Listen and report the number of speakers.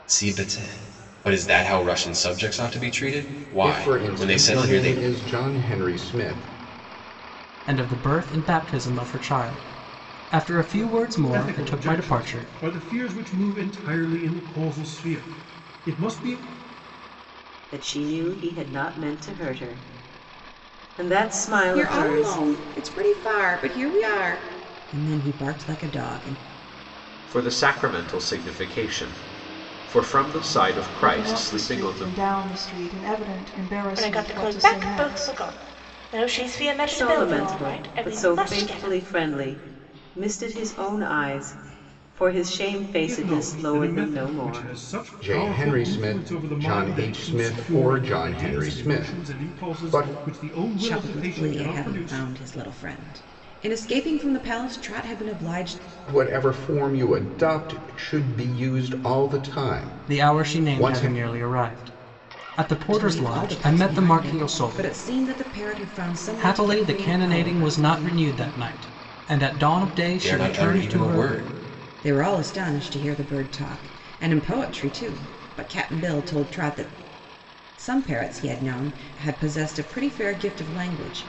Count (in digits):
9